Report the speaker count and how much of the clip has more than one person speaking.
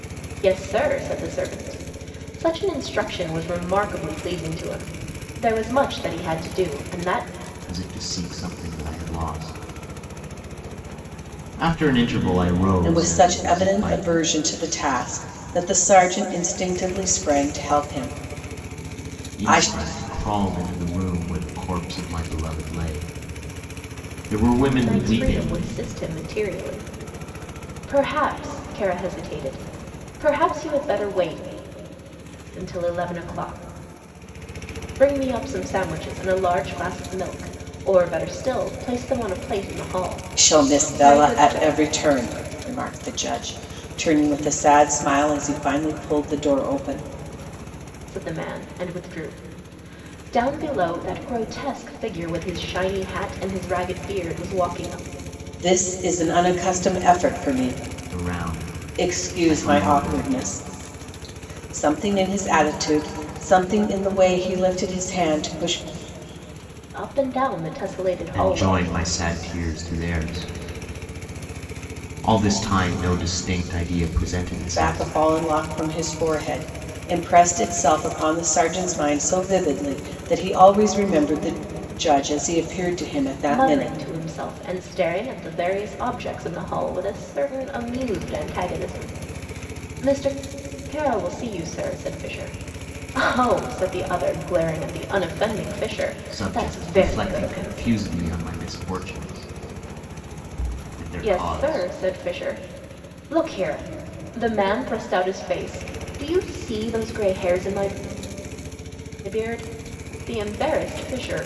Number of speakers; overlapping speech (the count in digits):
3, about 8%